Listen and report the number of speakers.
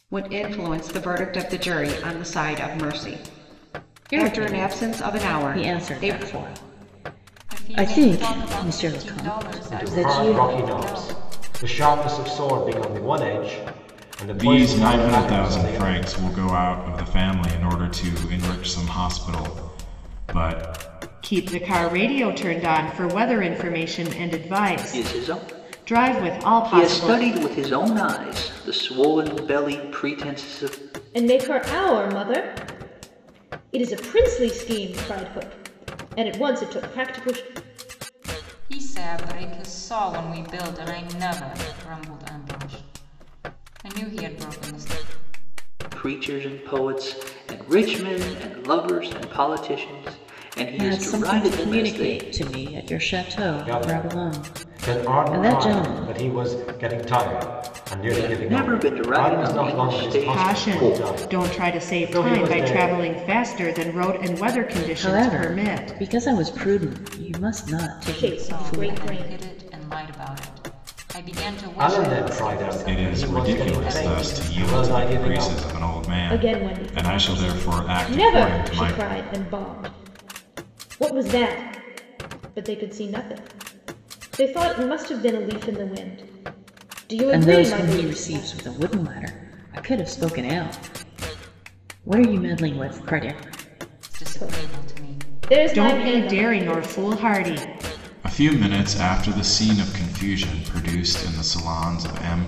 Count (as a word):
eight